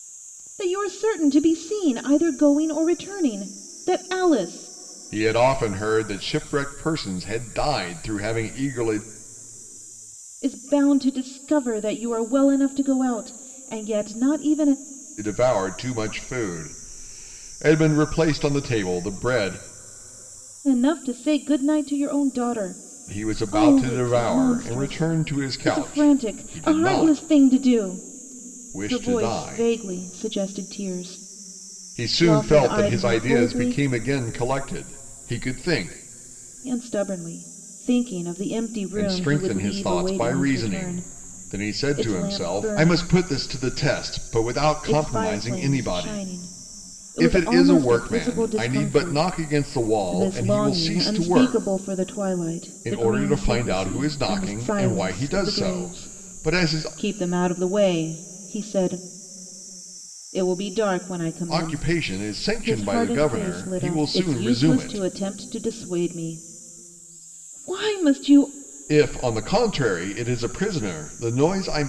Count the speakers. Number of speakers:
2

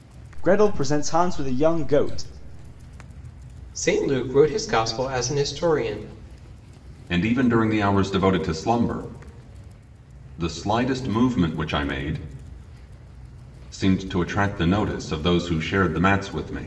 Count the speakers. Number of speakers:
3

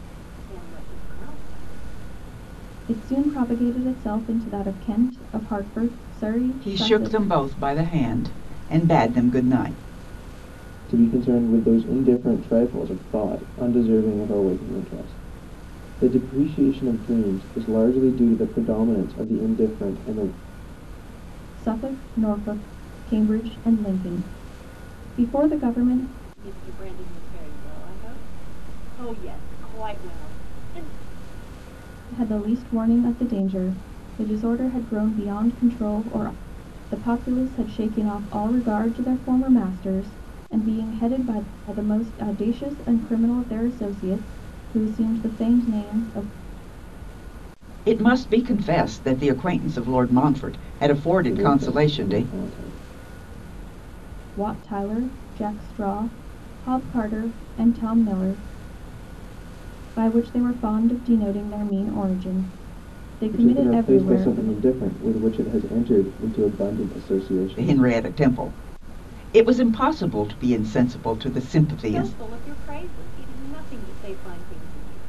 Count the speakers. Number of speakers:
4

